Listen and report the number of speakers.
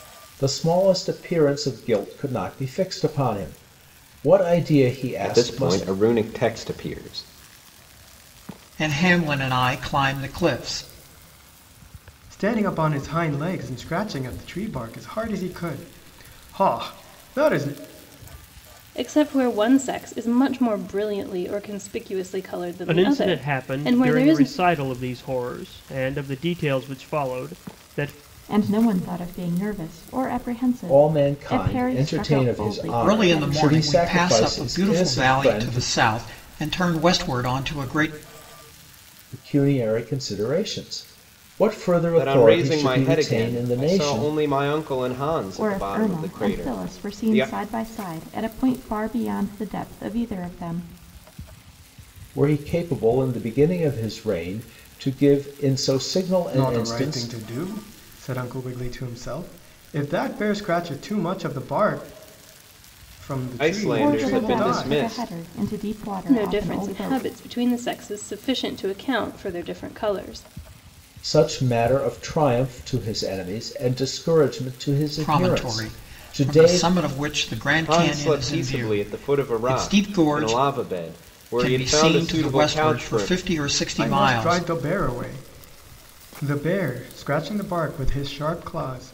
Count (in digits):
7